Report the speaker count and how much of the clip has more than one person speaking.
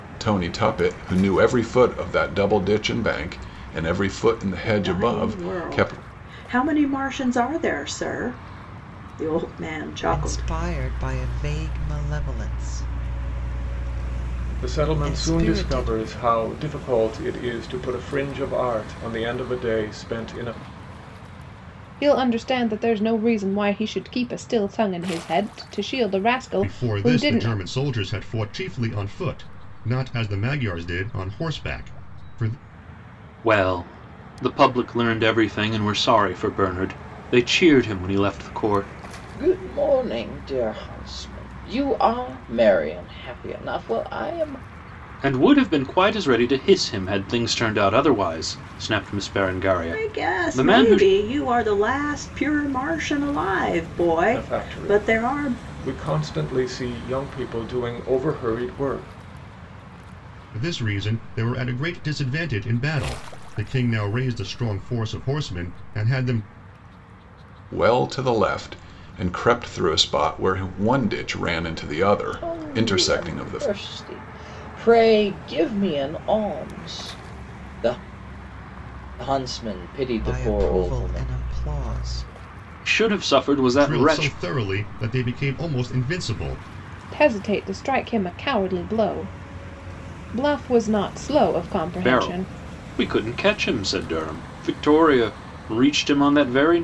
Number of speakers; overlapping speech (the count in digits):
8, about 11%